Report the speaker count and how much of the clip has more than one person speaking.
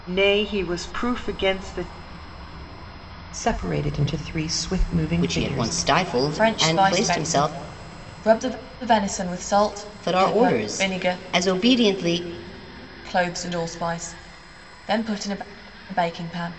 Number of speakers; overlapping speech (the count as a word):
four, about 19%